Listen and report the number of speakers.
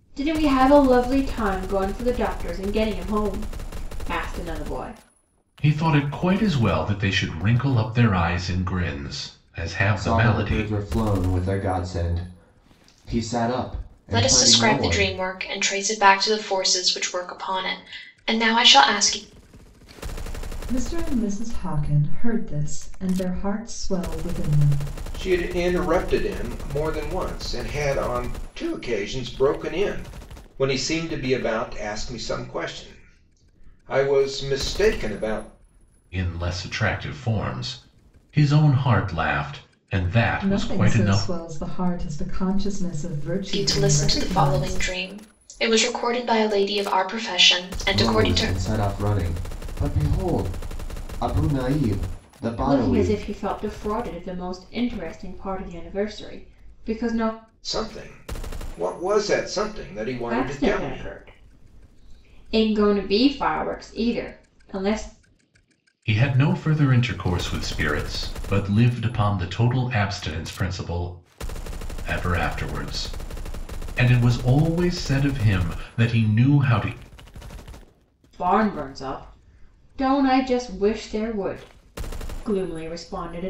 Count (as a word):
six